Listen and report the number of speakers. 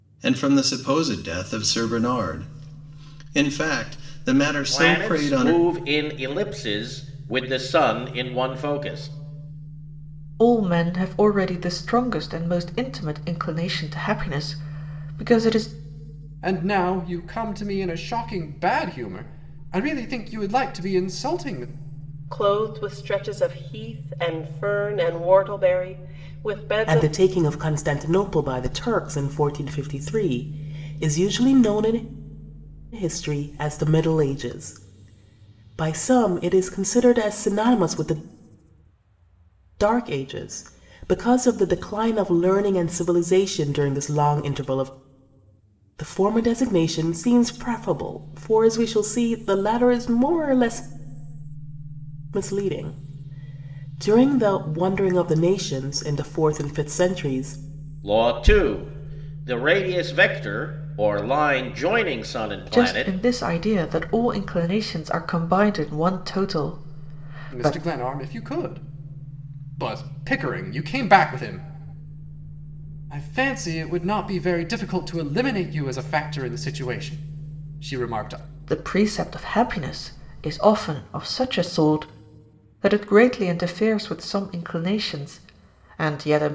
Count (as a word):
six